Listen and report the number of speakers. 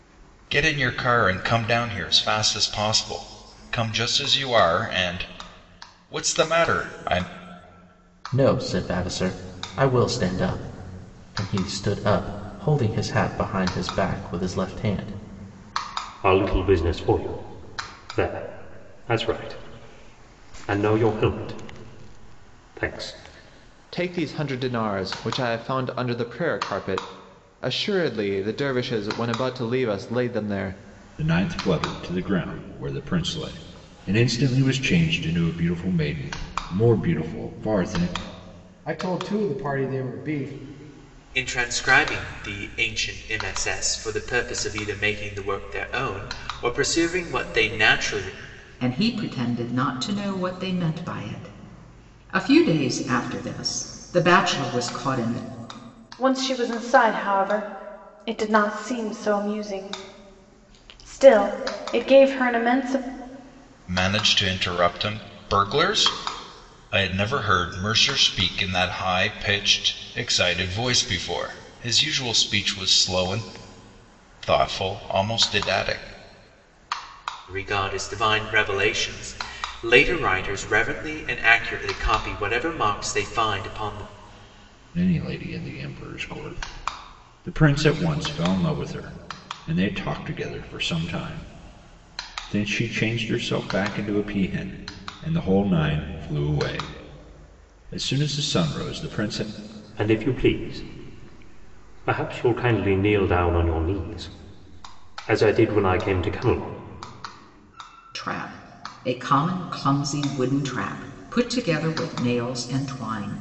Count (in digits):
9